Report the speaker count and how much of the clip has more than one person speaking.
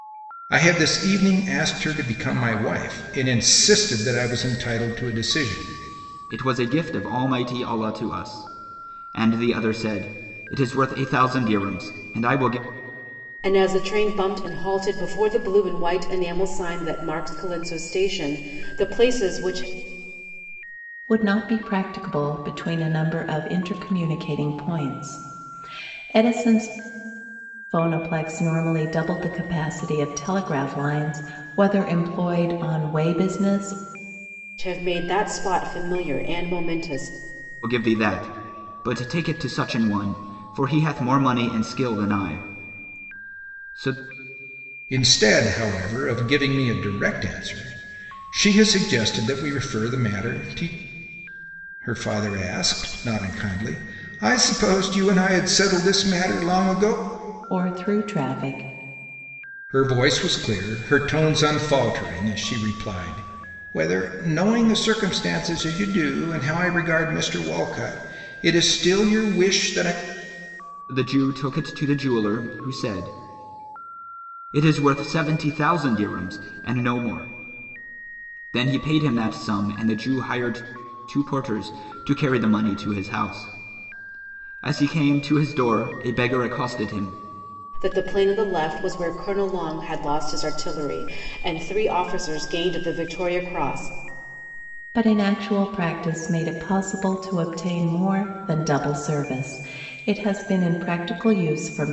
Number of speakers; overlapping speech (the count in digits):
4, no overlap